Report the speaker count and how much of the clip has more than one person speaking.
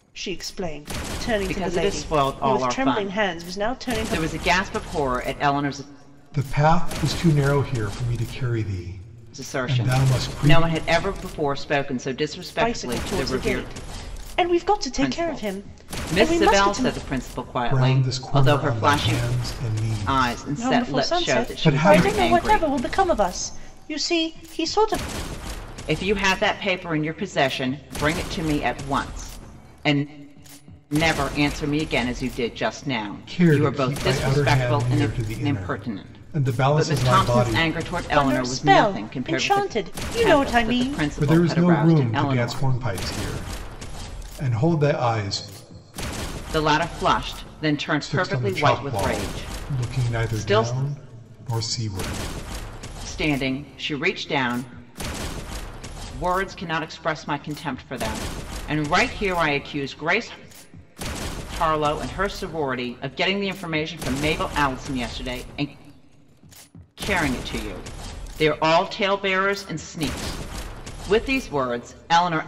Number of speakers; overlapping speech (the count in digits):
3, about 31%